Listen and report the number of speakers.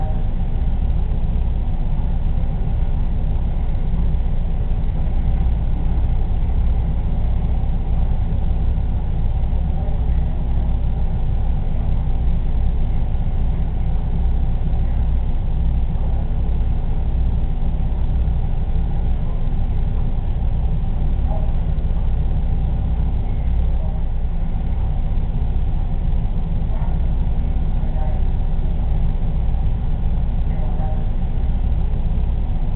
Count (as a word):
zero